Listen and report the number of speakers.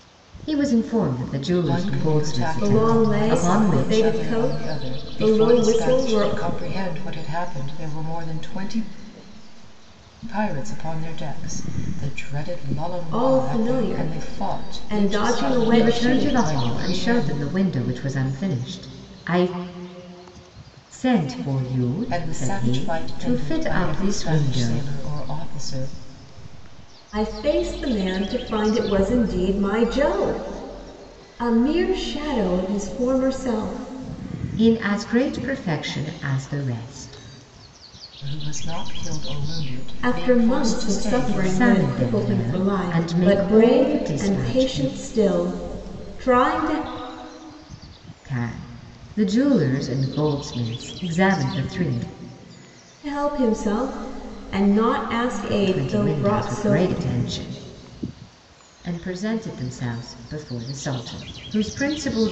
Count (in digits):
3